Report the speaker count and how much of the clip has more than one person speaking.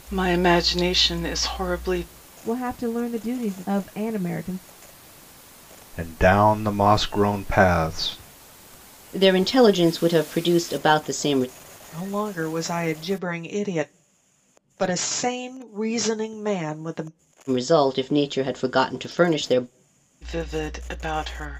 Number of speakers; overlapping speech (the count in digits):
5, no overlap